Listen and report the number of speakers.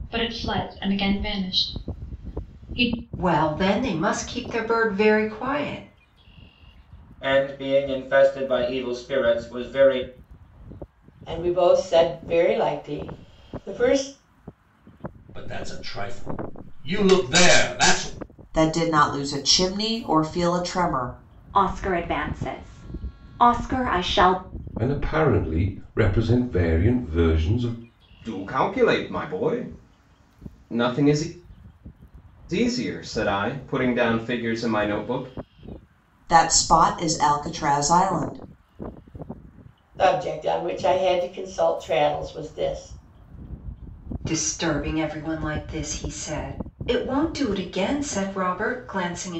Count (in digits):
9